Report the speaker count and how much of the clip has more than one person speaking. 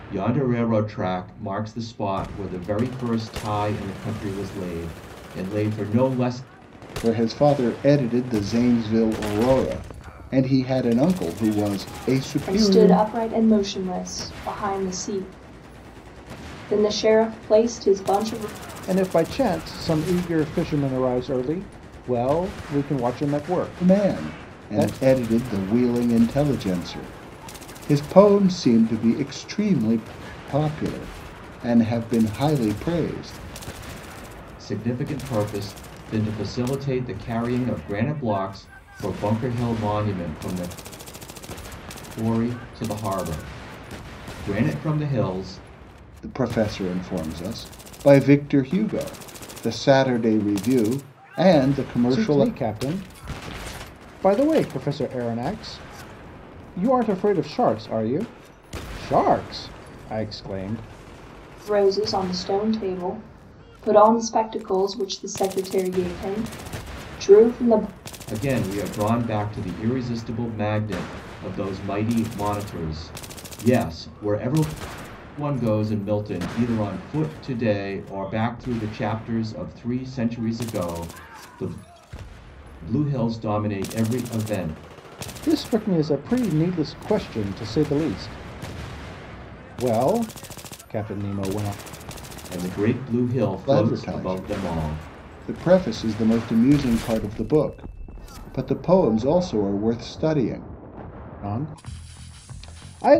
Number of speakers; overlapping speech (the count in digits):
4, about 3%